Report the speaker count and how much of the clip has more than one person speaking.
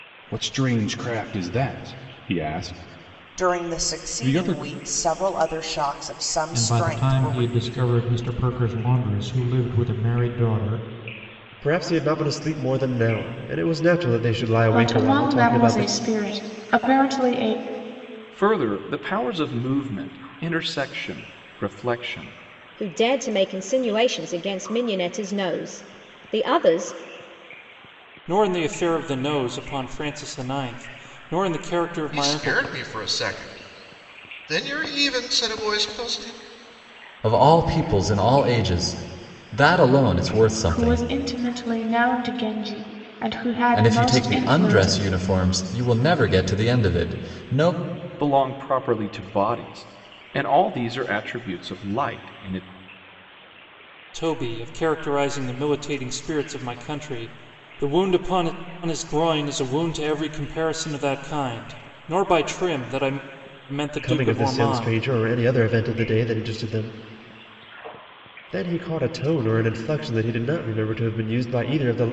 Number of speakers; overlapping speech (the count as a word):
ten, about 10%